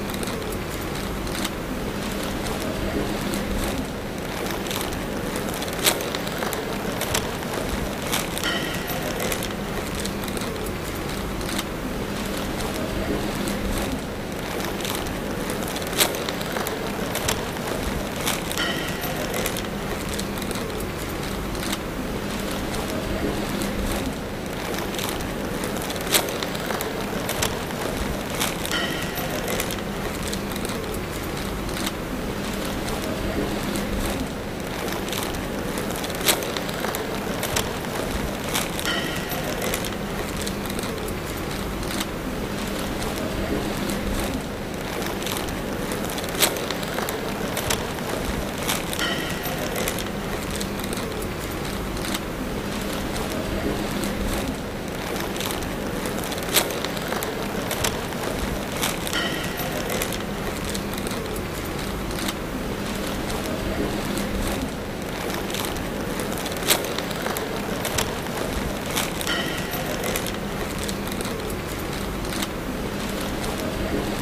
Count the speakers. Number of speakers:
0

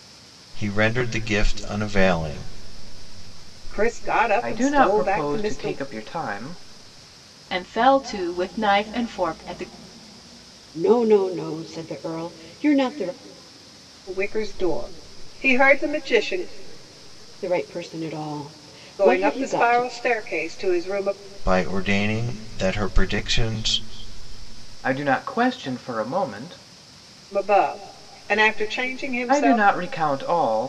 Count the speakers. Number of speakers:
5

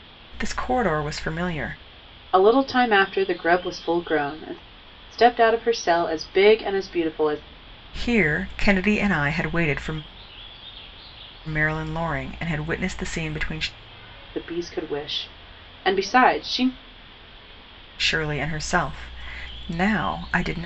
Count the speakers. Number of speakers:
2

